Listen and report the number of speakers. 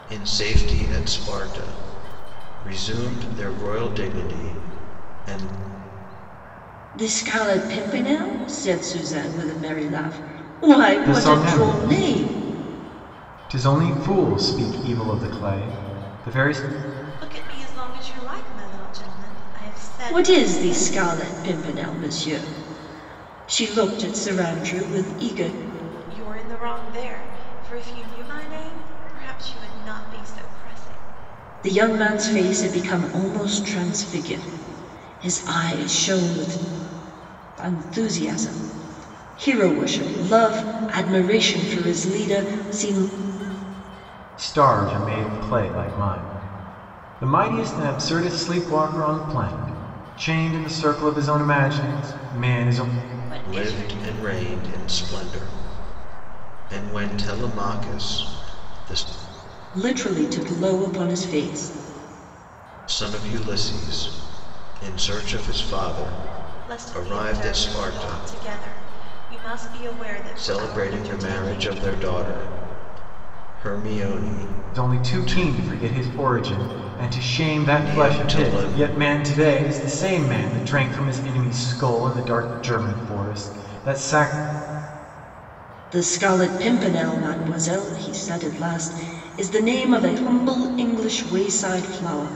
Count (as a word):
four